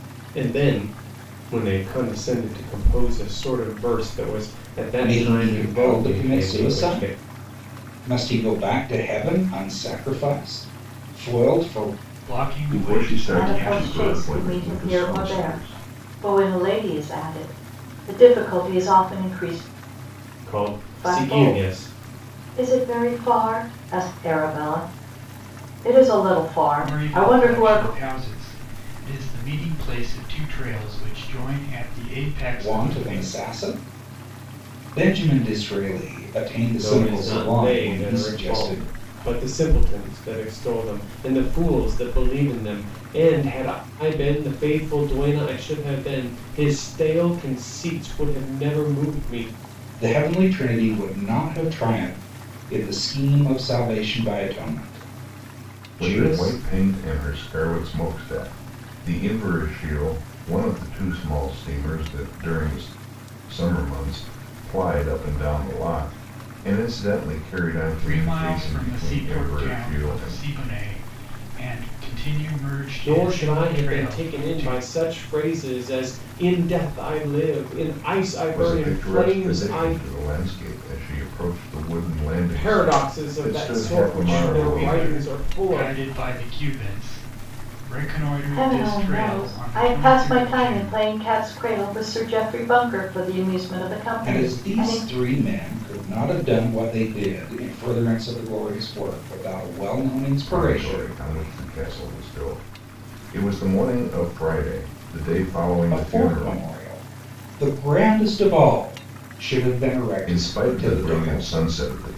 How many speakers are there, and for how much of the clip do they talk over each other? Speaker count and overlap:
5, about 24%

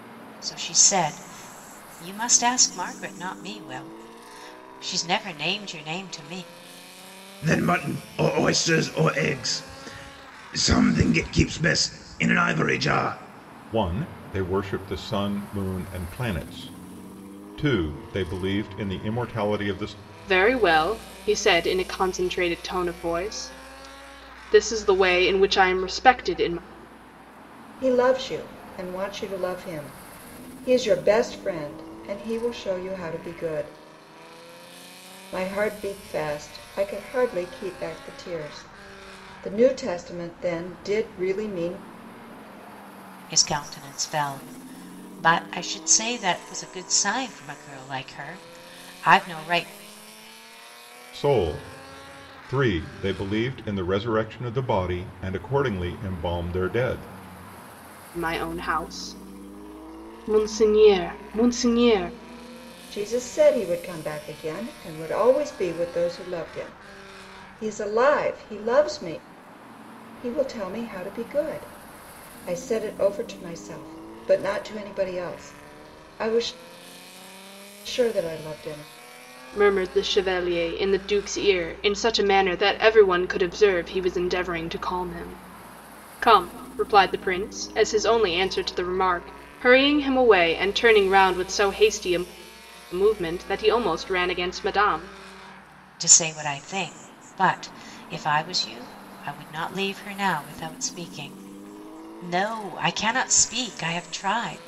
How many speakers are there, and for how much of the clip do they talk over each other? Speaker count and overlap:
5, no overlap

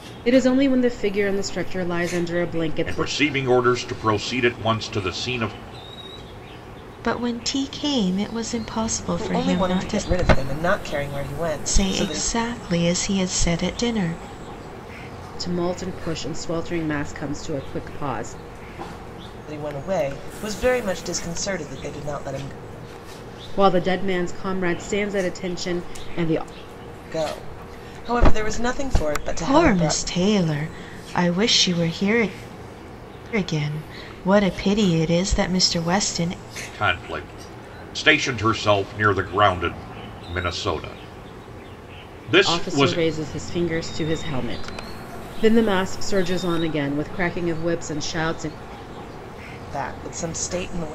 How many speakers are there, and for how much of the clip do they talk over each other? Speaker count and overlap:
4, about 6%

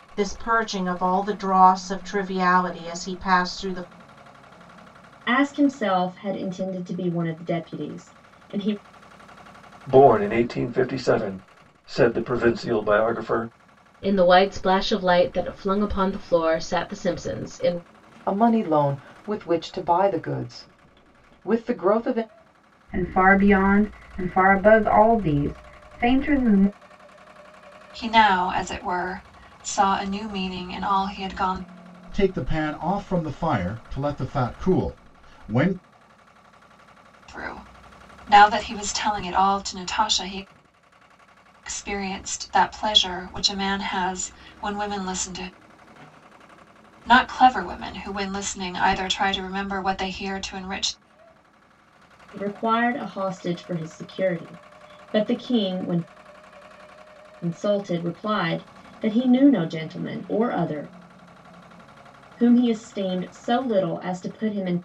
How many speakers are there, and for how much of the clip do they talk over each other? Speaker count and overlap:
8, no overlap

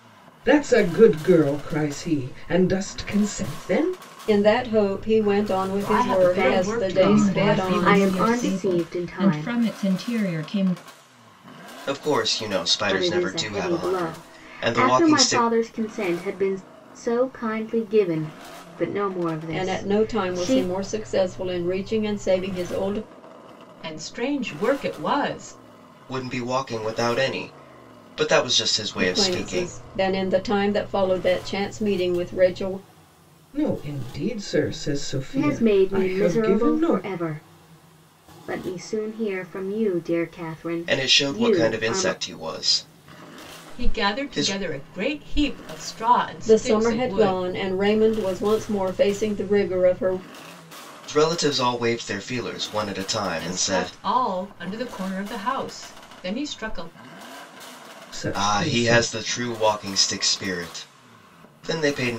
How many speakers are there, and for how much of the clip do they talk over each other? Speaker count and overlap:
6, about 24%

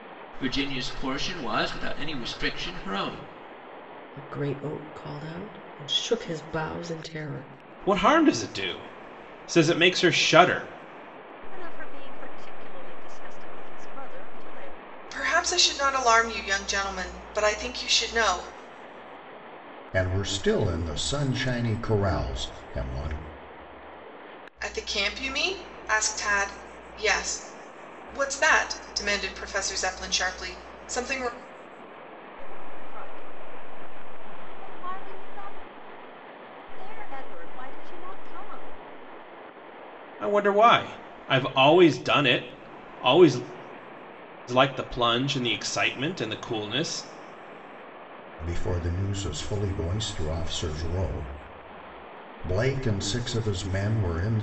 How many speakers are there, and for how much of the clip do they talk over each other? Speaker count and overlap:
6, no overlap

